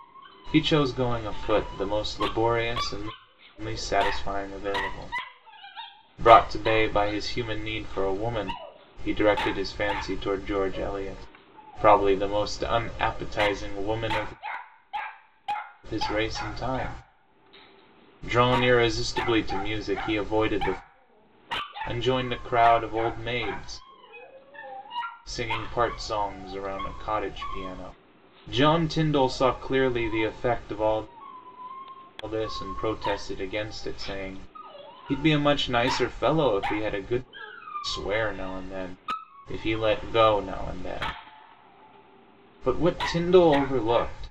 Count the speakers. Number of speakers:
1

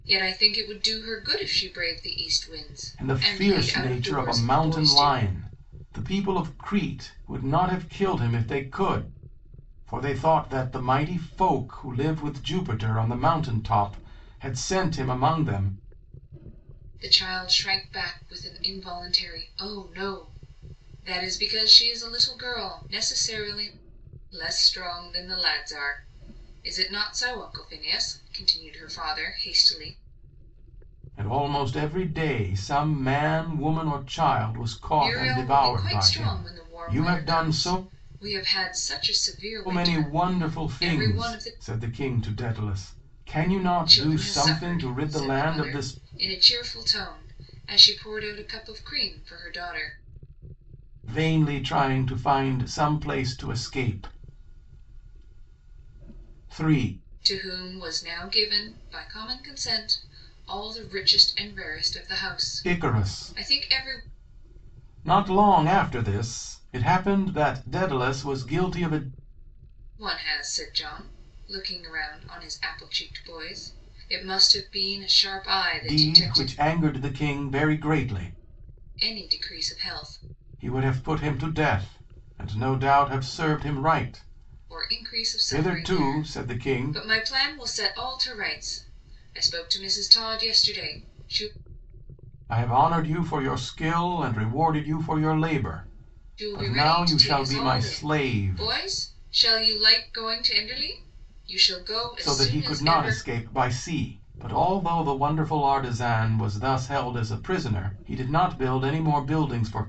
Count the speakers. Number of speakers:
2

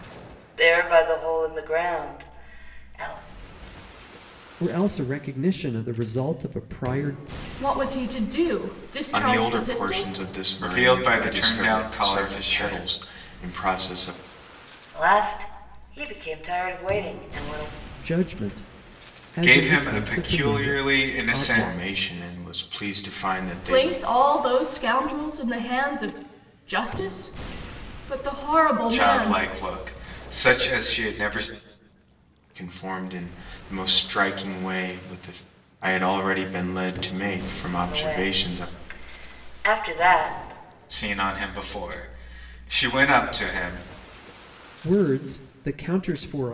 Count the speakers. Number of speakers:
5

